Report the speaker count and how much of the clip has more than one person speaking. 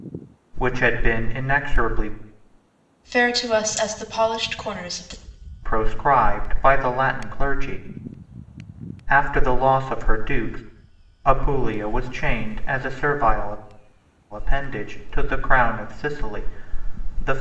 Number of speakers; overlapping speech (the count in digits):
2, no overlap